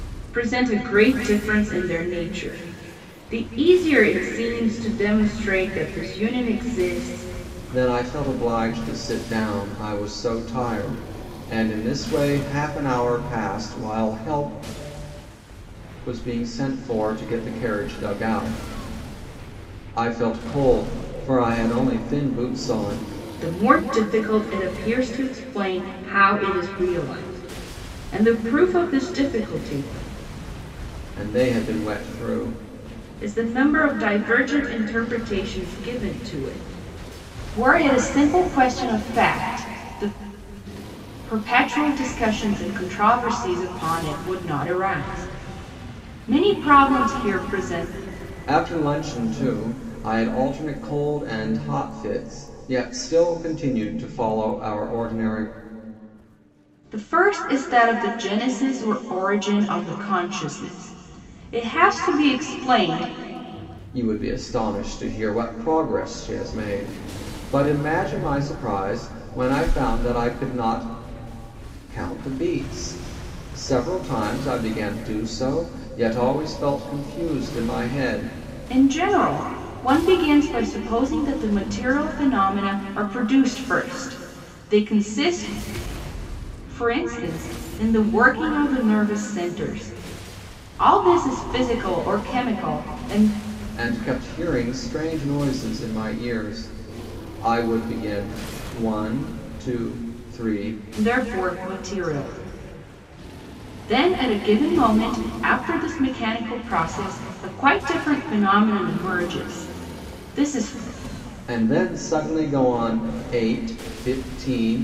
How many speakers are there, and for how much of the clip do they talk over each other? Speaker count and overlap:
2, no overlap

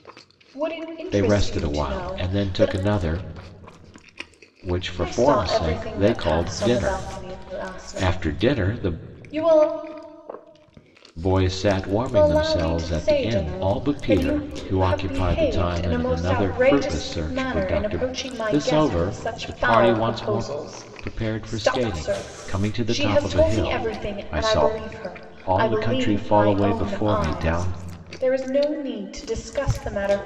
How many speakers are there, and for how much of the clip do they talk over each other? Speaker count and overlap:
2, about 63%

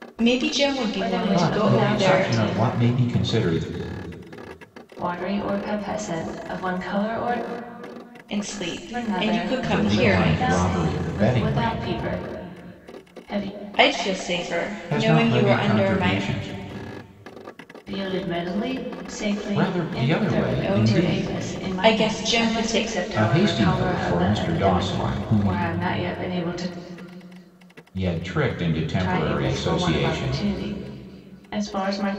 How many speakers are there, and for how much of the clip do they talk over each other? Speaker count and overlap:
3, about 42%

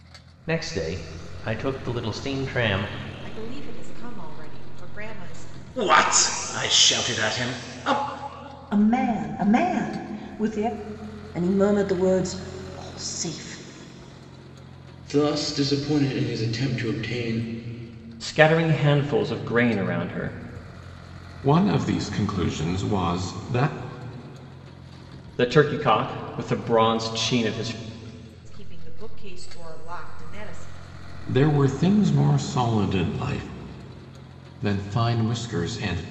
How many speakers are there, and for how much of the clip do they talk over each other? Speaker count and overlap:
8, no overlap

